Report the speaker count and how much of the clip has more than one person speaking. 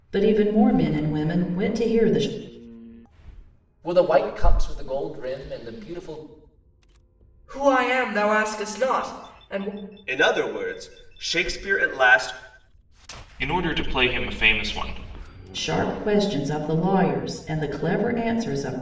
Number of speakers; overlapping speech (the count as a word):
five, no overlap